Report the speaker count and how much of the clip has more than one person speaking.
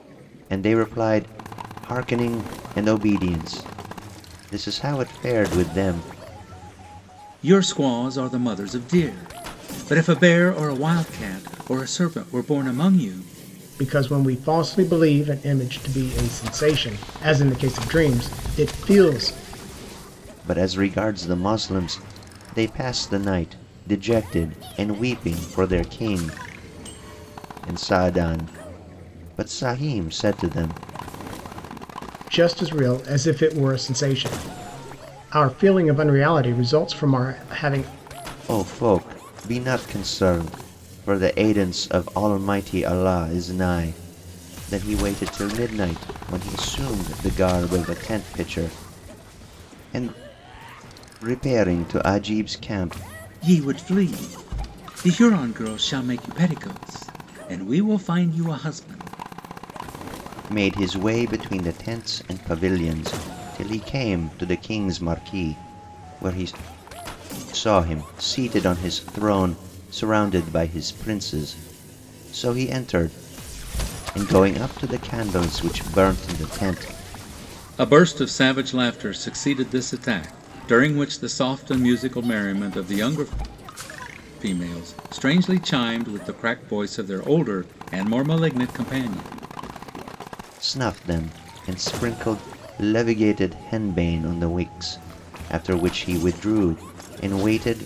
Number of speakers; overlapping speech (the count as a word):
three, no overlap